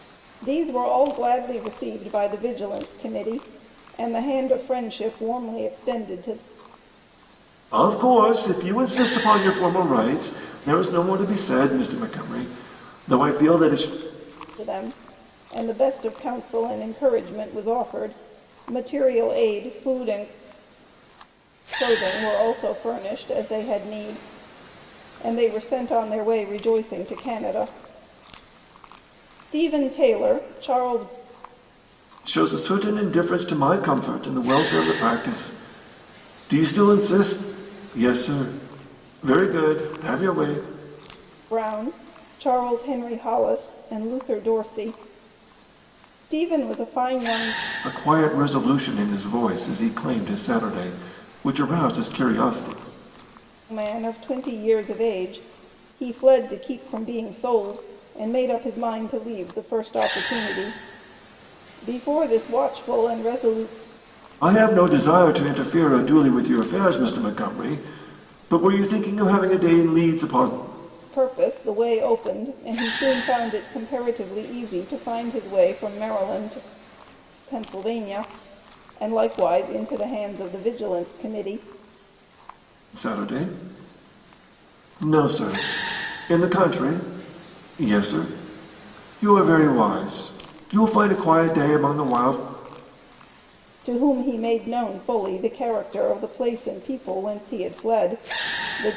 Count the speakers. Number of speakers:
two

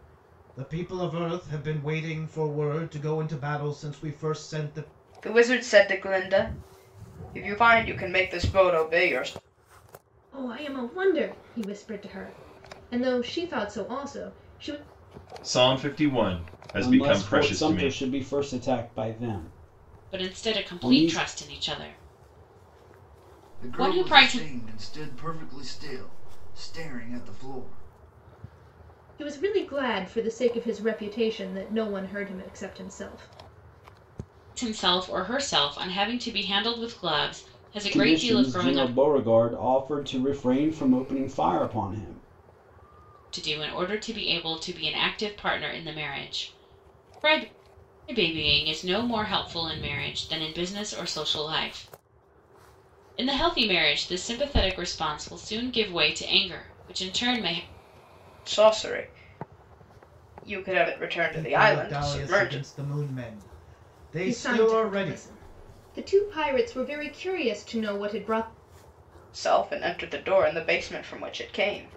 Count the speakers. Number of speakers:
seven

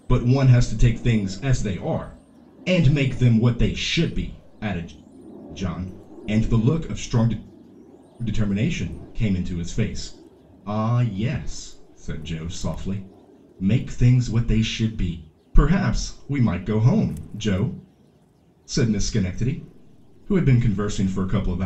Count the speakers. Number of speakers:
one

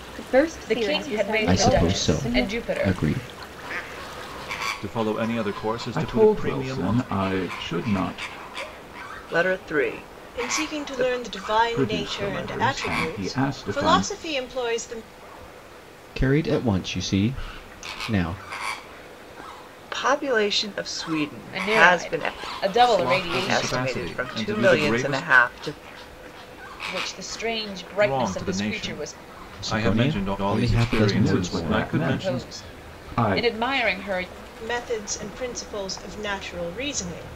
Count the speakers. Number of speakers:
seven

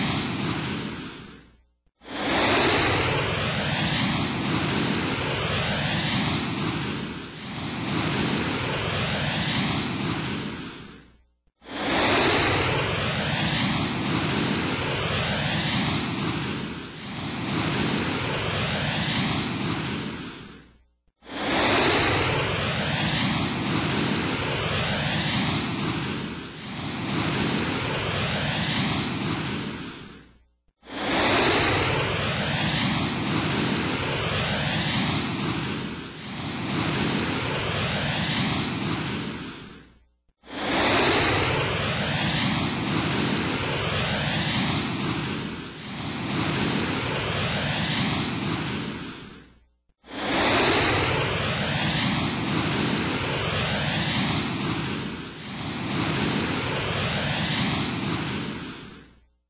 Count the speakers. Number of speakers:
zero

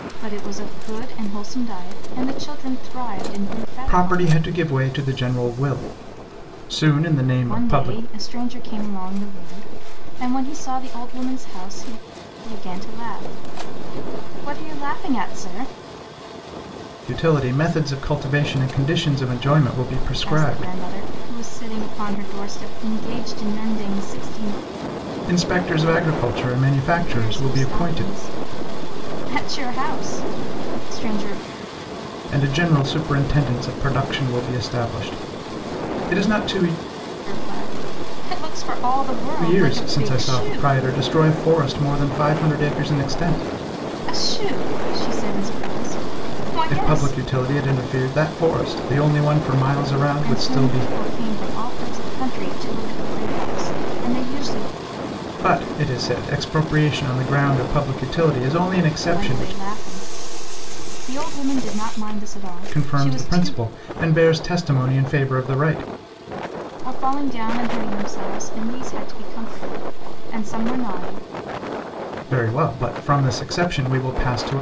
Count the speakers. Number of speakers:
two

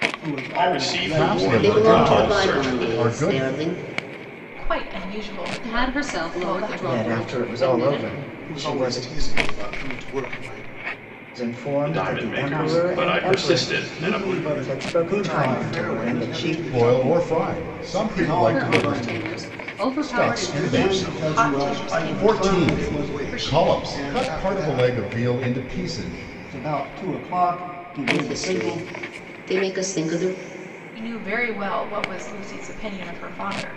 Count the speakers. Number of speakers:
eight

